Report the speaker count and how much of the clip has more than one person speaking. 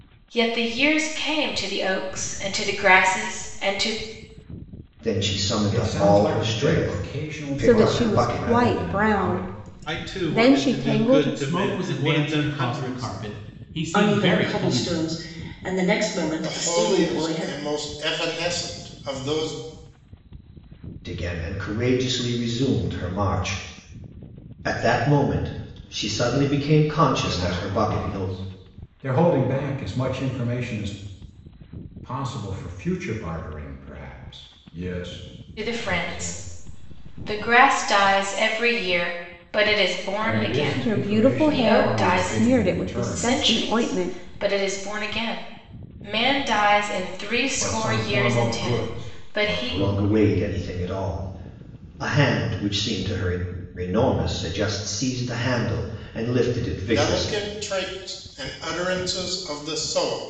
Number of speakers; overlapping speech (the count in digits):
8, about 31%